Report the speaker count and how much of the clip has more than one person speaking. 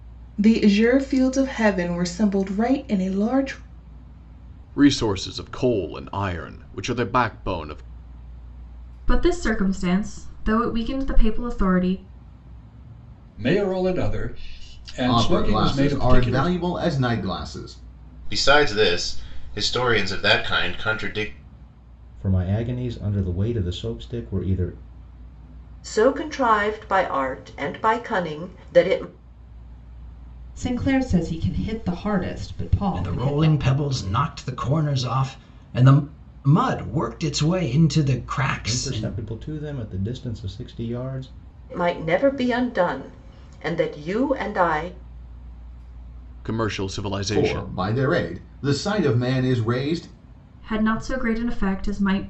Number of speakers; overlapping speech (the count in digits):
10, about 6%